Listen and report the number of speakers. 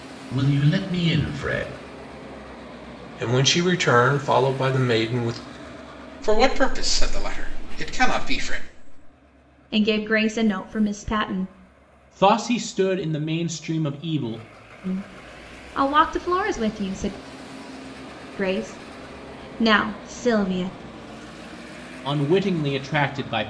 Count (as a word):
five